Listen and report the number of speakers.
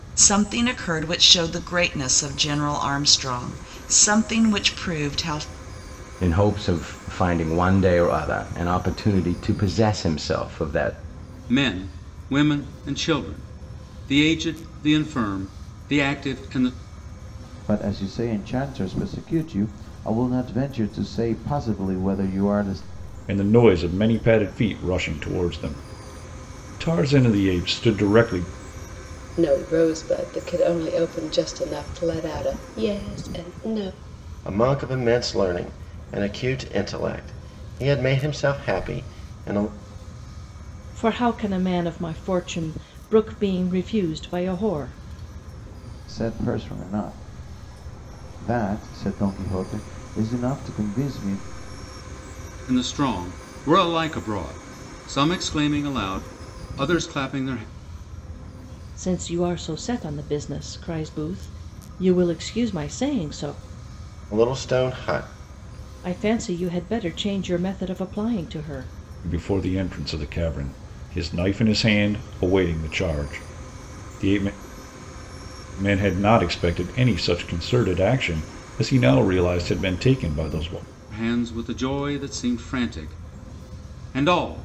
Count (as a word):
eight